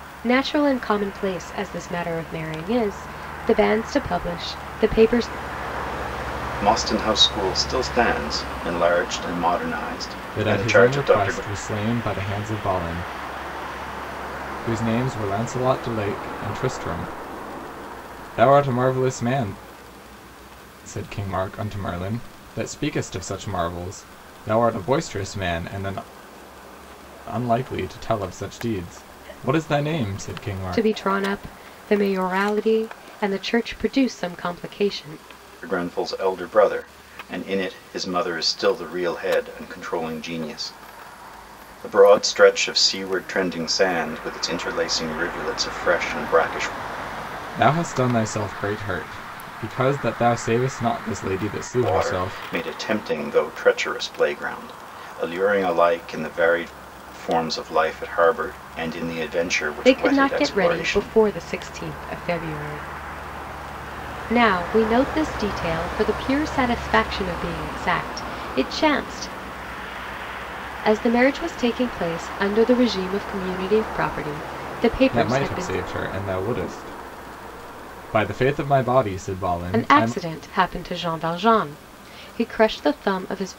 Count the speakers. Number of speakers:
3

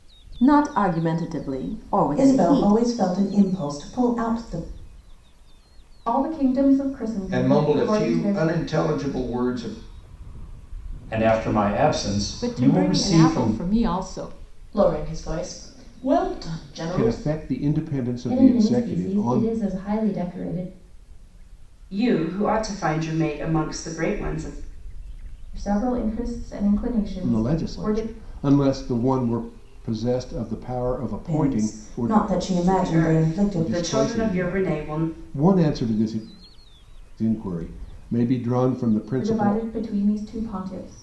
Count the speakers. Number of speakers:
10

